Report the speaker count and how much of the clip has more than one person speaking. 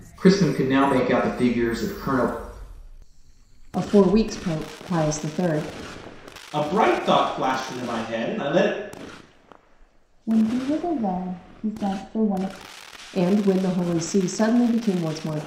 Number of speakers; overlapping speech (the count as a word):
four, no overlap